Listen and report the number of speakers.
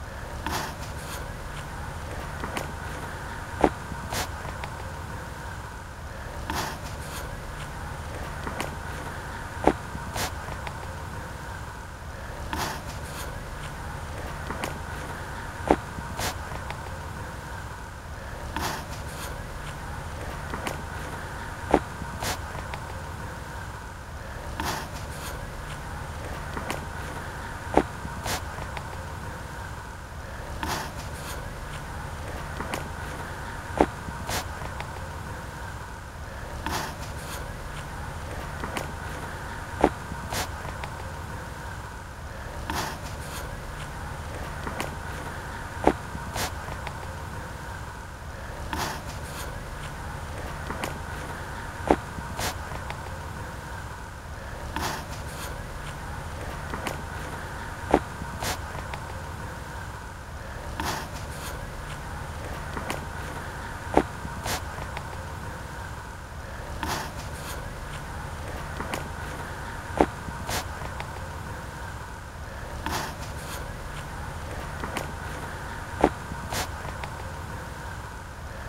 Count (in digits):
0